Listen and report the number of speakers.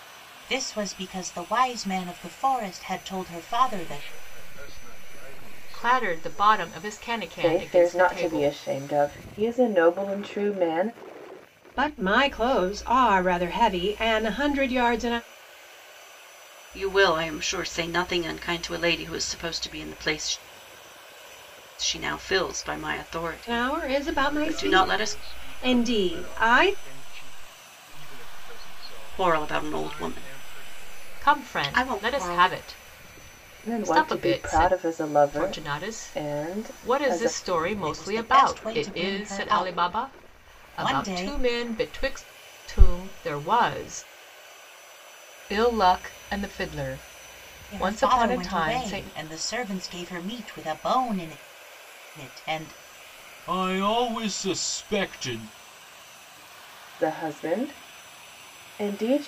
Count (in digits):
6